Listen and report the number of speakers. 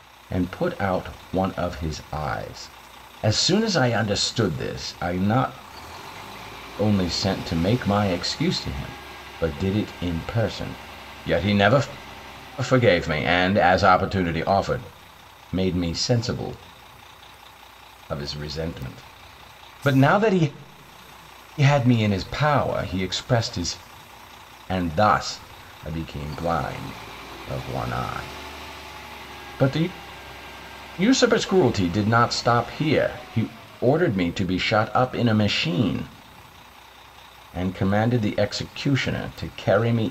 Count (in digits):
1